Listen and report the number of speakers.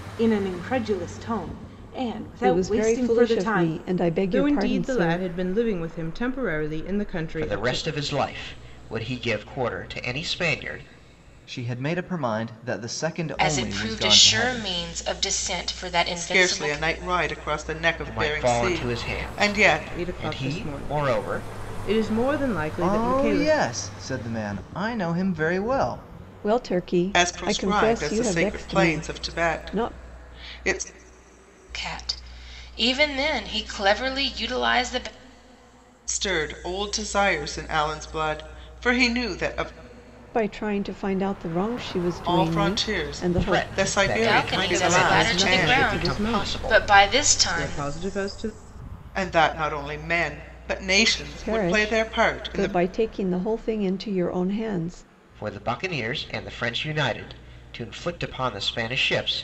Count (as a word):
seven